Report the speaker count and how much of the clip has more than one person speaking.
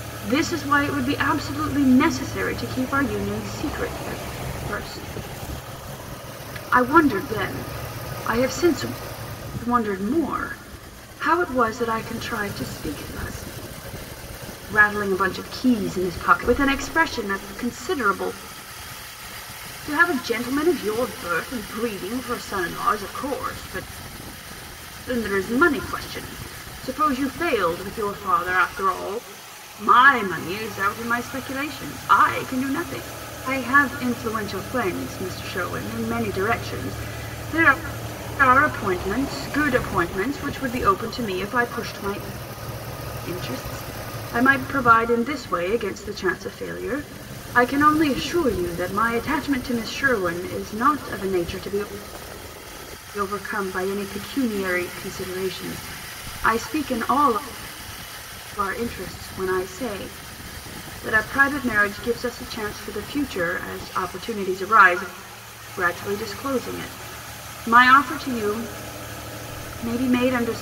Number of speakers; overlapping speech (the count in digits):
1, no overlap